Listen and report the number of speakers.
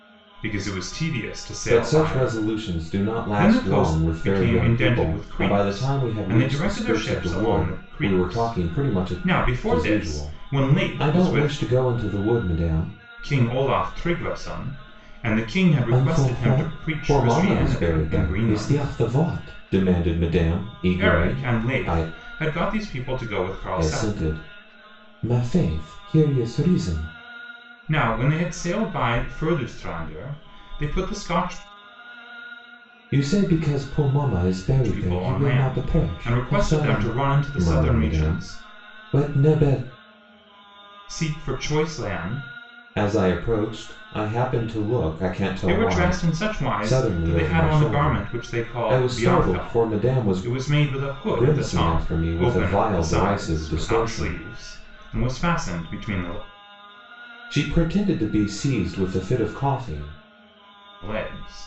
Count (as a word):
two